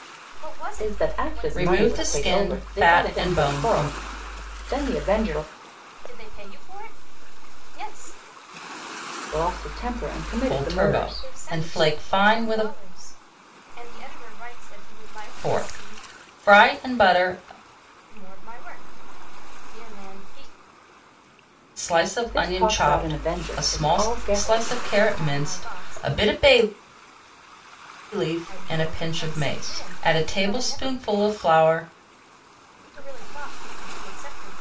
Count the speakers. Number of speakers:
3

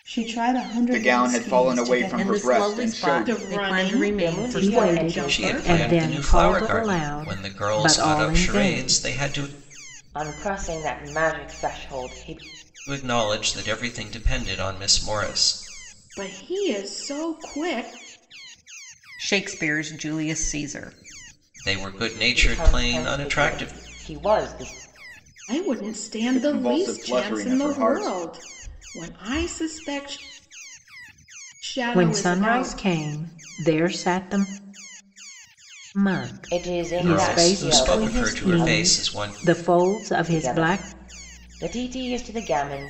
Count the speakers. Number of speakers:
7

